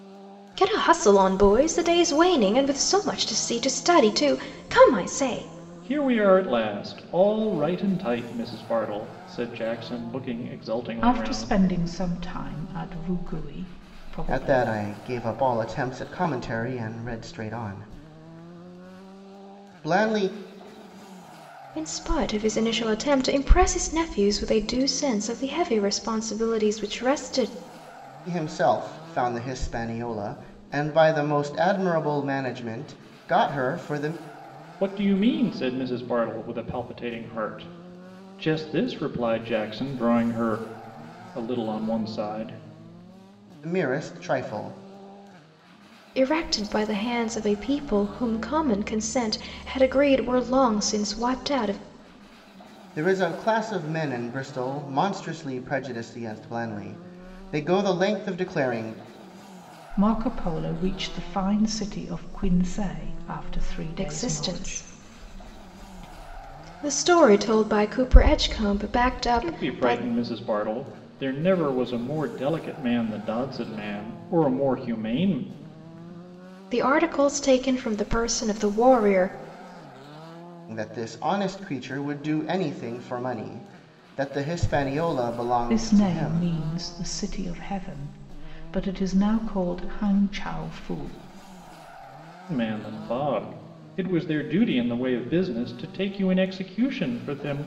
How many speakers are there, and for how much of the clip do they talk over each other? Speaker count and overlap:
4, about 3%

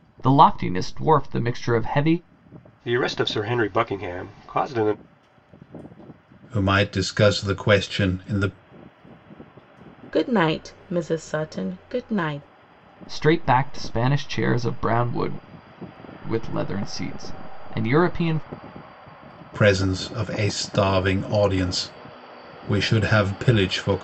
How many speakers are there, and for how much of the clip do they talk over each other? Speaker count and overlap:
4, no overlap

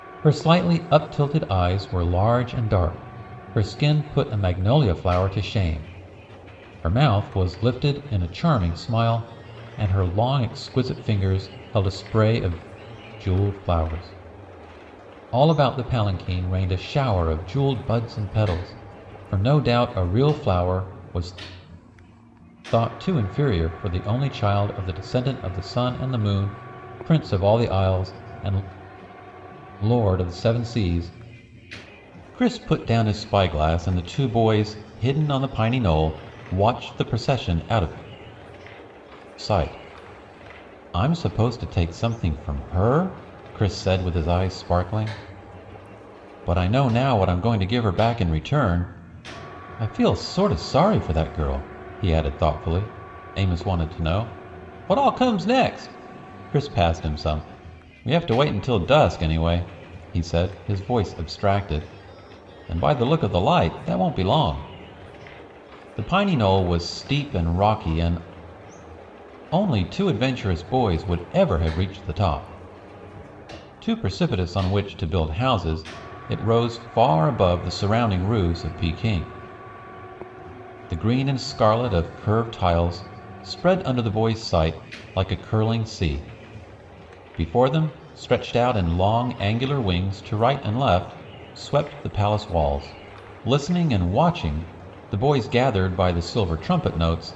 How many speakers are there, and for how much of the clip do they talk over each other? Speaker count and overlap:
1, no overlap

